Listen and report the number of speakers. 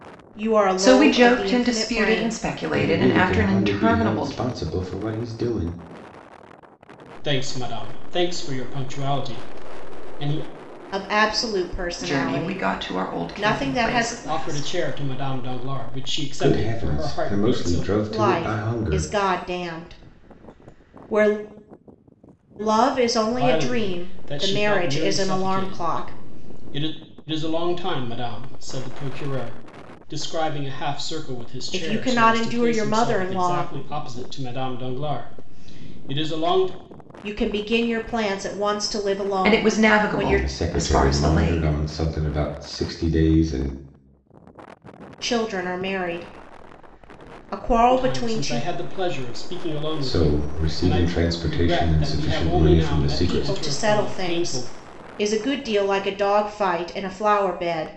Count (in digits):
4